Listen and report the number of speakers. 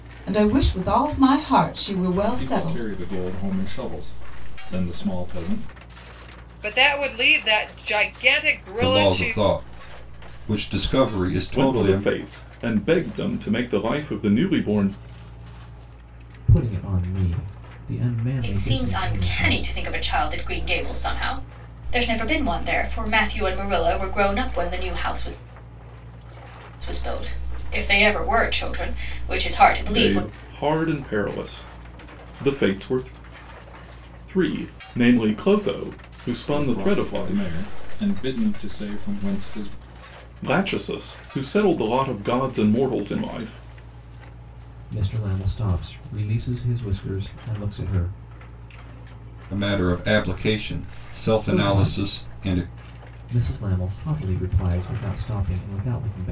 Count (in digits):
7